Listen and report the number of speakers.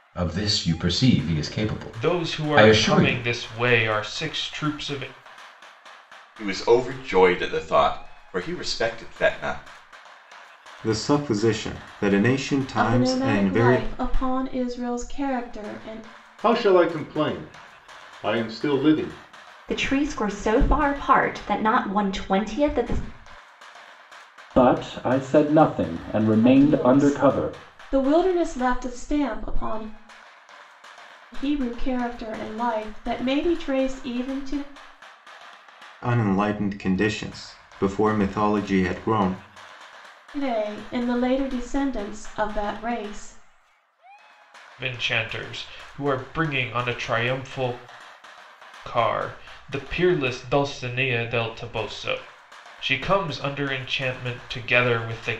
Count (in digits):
8